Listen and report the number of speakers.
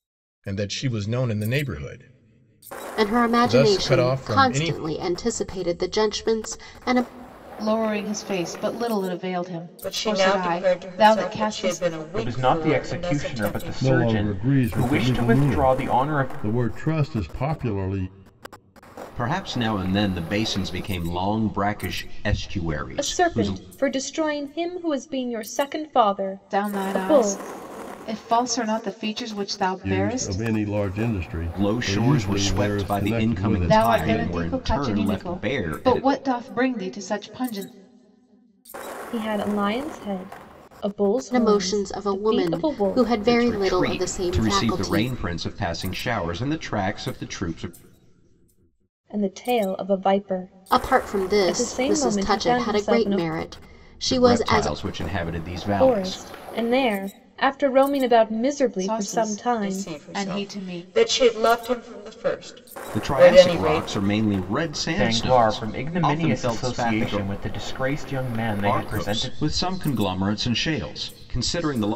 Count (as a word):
eight